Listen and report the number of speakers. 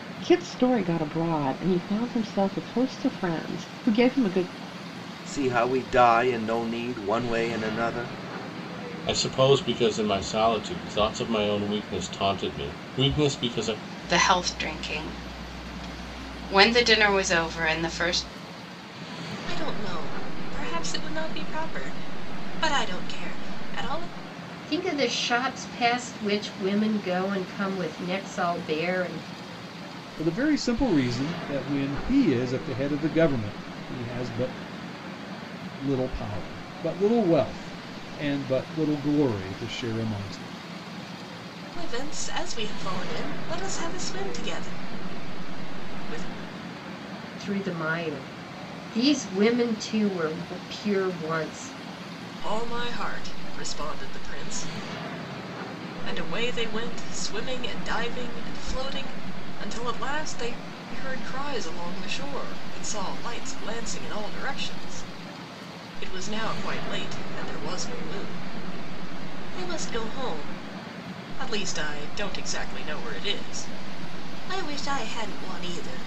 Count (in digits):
7